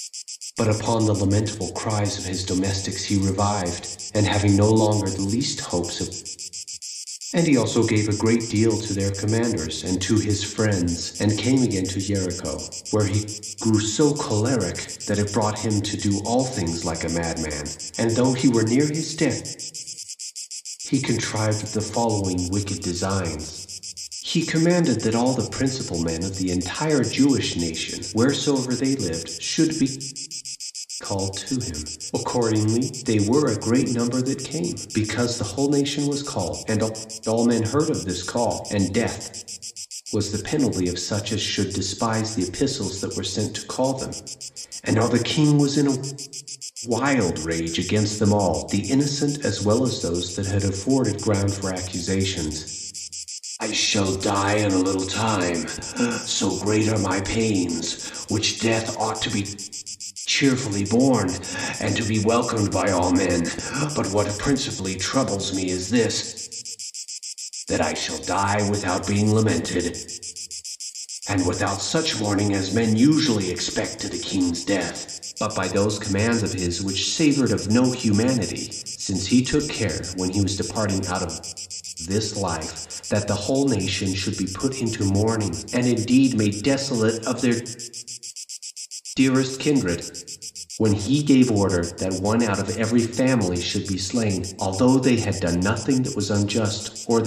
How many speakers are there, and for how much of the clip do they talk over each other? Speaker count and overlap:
1, no overlap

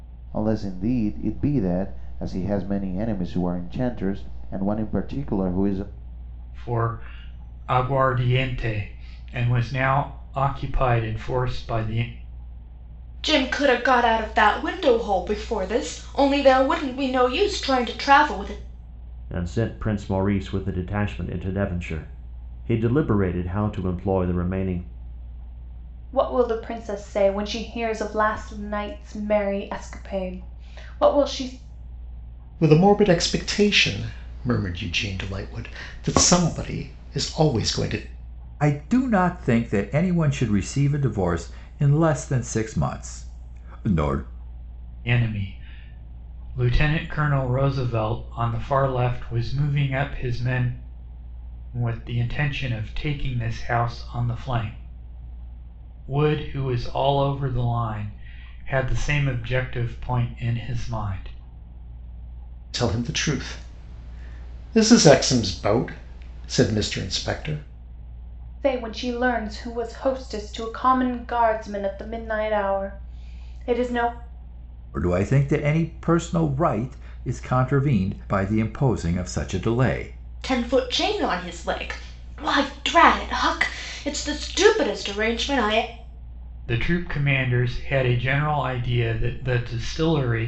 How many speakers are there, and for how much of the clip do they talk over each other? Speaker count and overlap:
7, no overlap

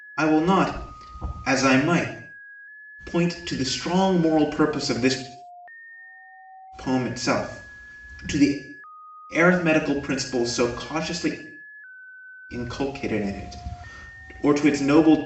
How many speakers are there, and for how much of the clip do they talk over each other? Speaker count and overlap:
1, no overlap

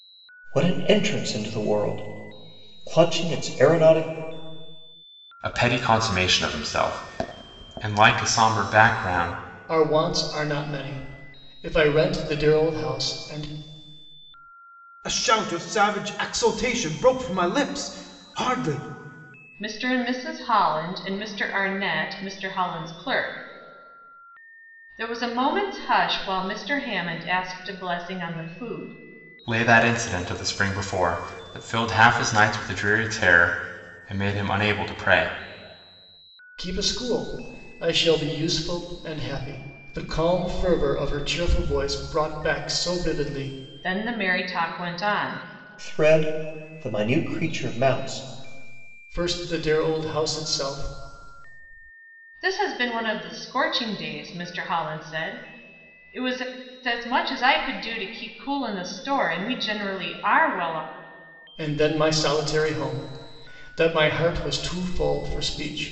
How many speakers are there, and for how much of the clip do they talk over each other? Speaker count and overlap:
5, no overlap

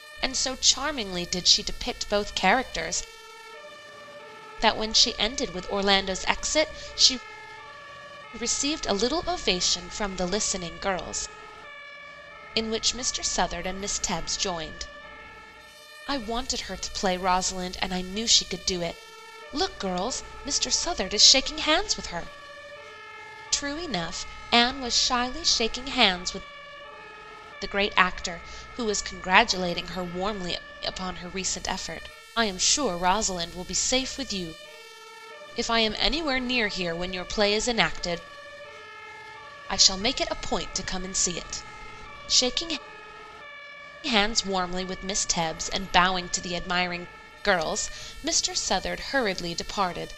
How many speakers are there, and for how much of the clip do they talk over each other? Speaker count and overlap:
1, no overlap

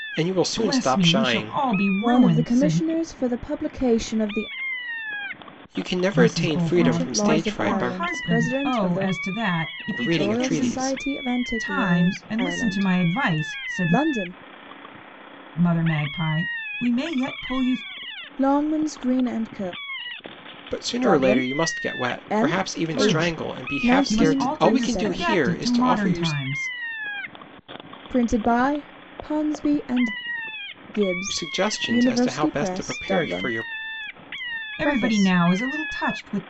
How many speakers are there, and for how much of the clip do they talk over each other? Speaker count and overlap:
3, about 46%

